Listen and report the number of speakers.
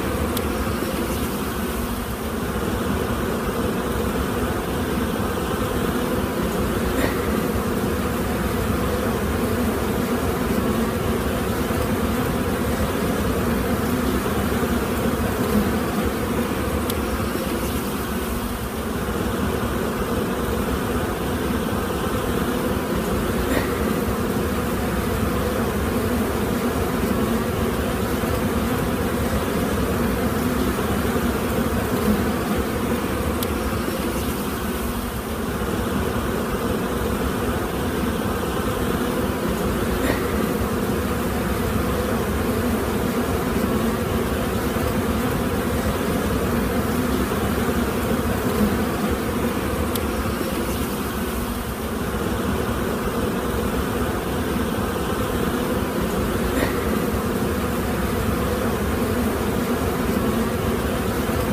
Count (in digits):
0